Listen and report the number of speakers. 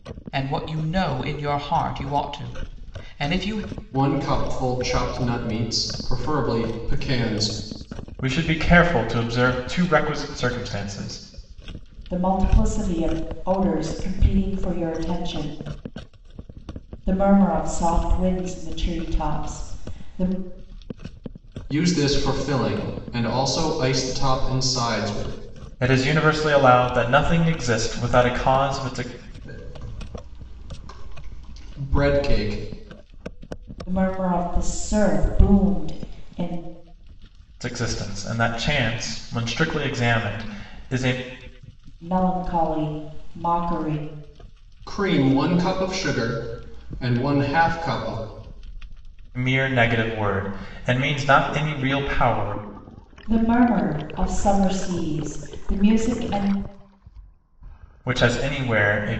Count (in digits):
4